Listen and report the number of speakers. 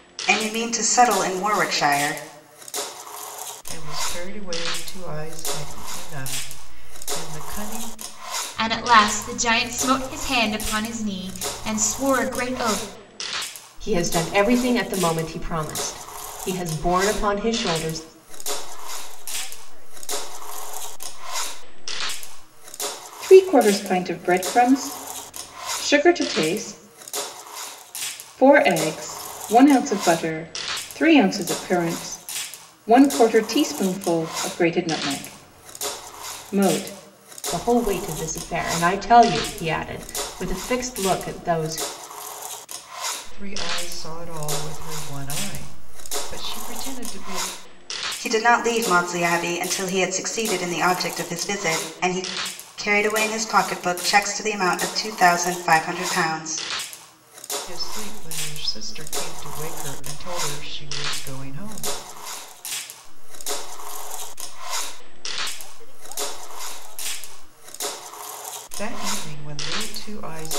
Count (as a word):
six